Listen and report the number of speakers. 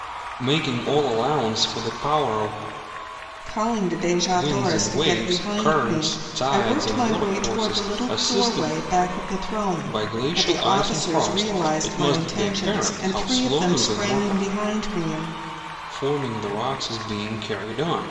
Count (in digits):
2